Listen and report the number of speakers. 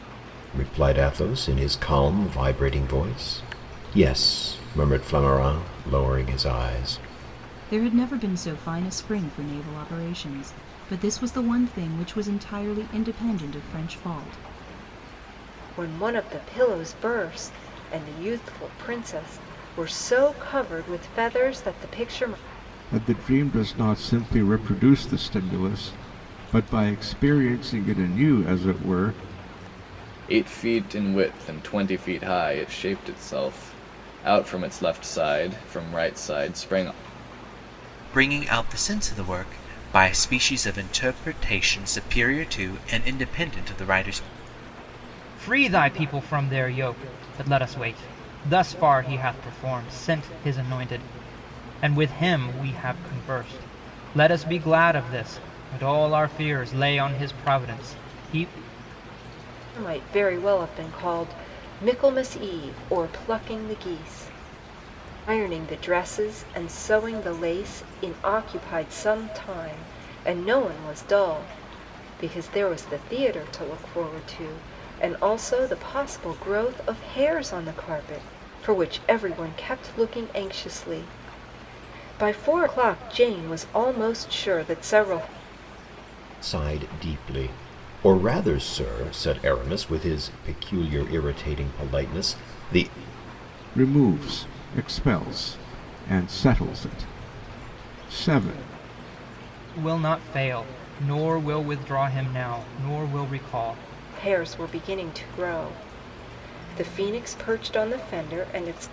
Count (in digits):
7